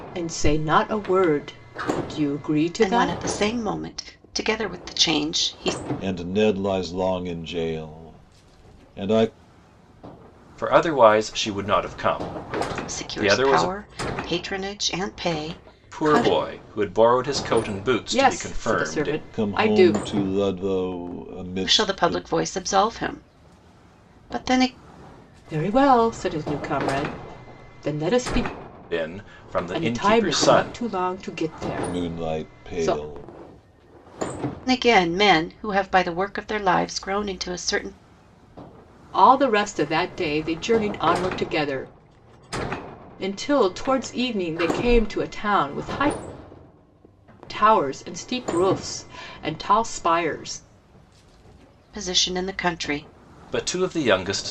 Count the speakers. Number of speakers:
4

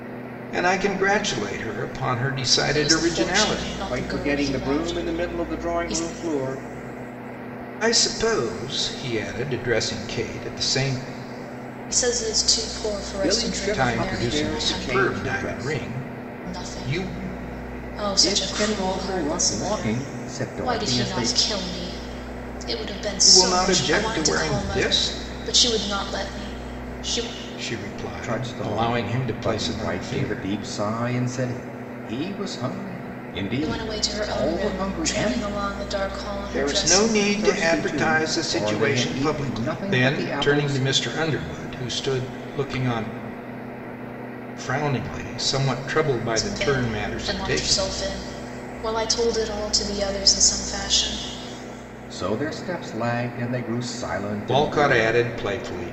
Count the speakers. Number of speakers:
3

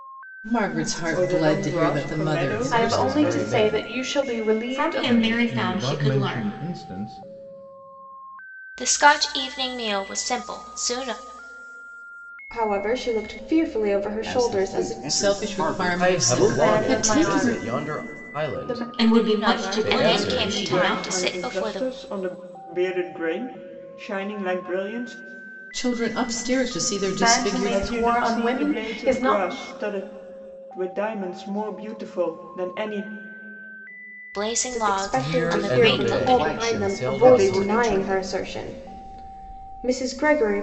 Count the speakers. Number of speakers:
9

